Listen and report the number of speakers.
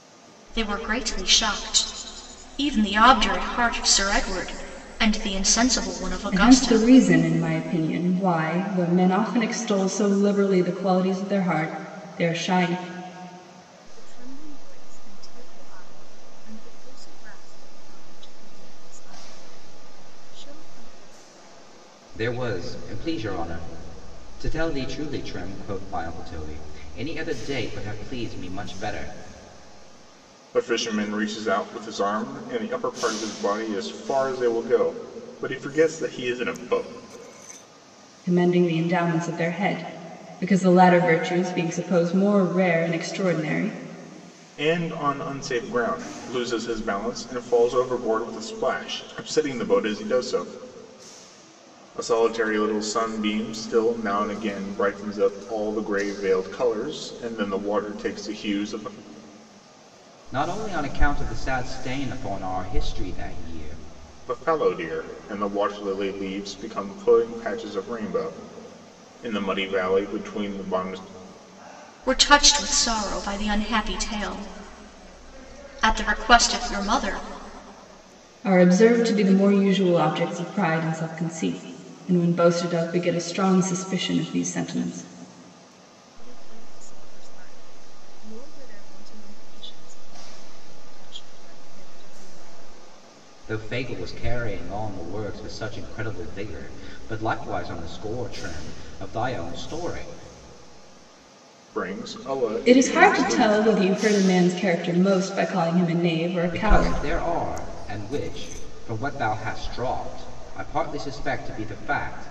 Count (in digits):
5